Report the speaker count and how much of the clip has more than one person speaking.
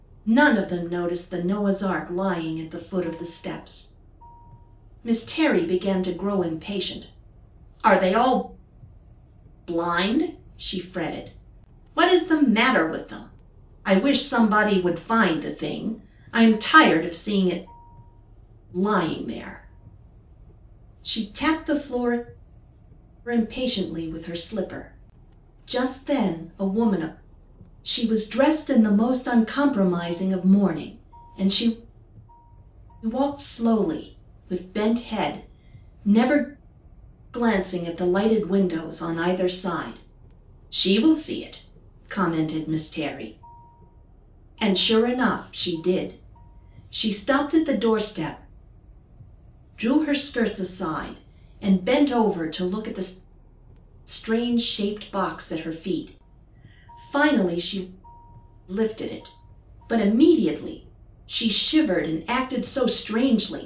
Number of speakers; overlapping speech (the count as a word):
one, no overlap